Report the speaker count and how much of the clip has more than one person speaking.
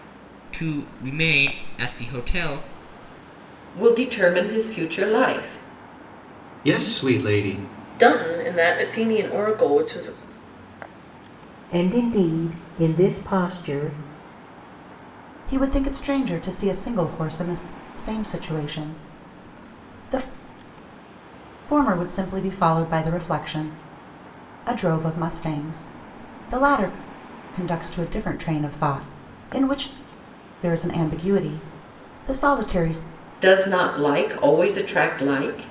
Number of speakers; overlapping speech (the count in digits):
6, no overlap